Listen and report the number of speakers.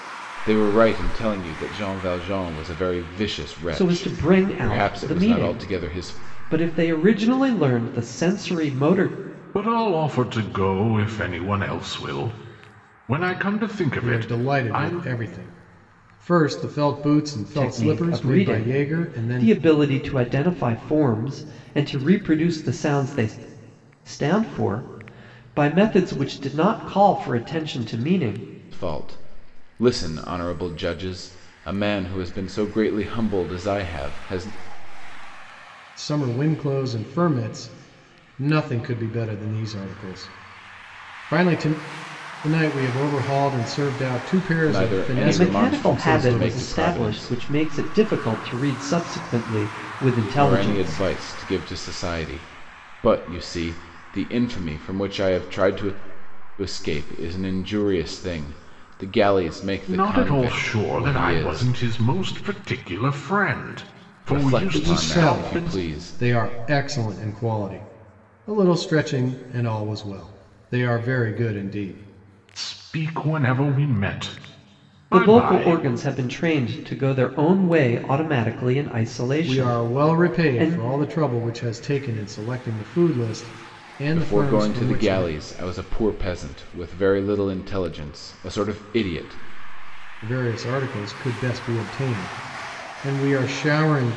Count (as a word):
four